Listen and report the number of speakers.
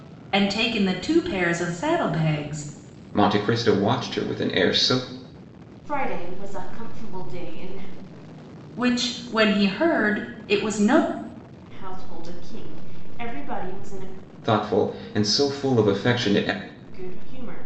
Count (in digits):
3